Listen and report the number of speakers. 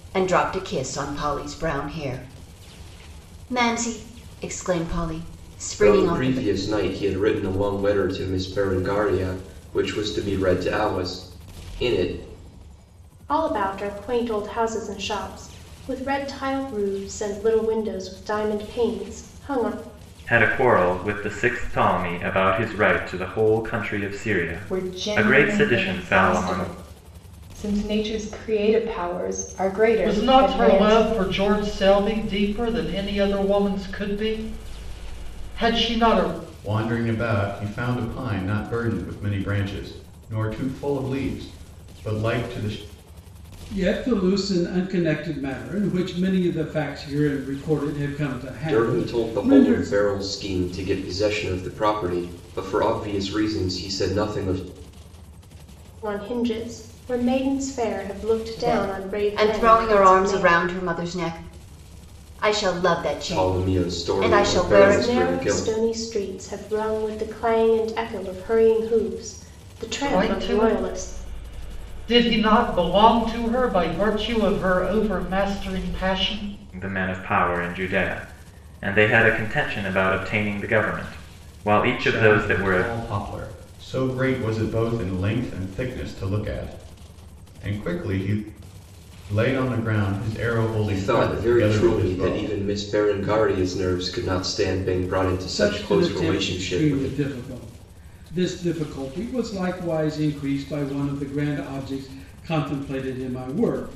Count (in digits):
8